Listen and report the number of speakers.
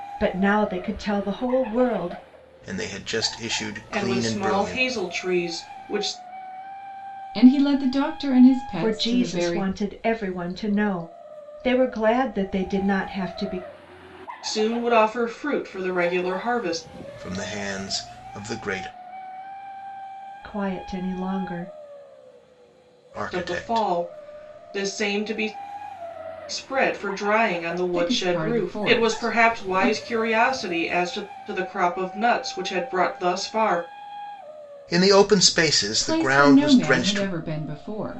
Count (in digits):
4